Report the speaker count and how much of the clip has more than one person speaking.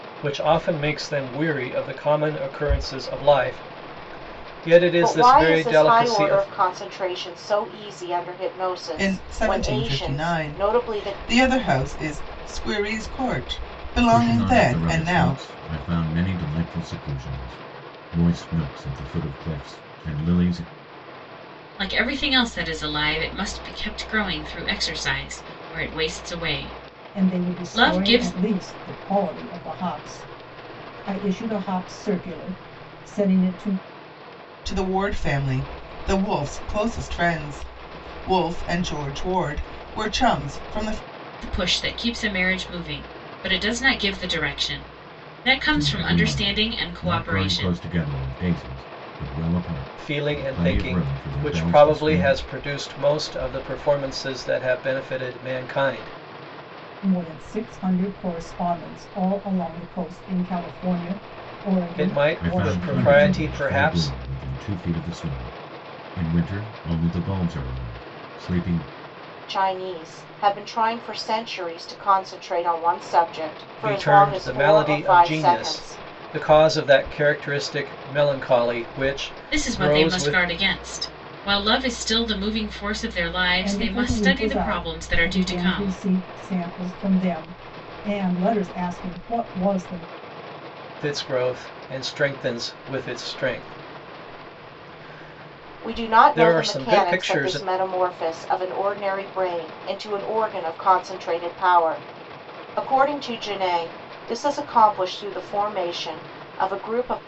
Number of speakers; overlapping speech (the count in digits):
6, about 19%